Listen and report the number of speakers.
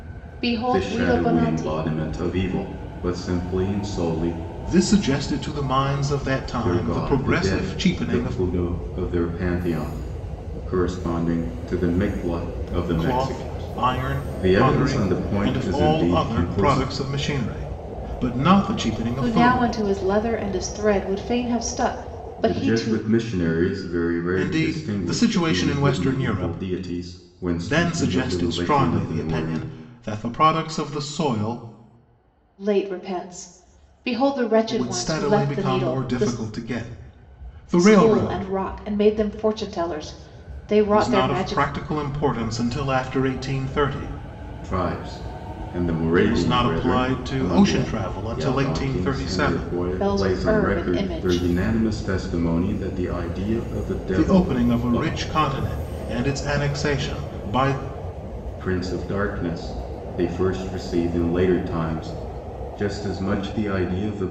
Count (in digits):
3